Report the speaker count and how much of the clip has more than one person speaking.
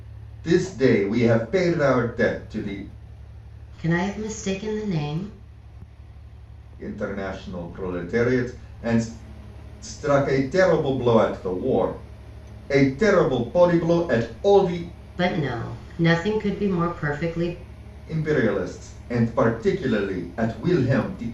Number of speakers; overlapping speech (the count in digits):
2, no overlap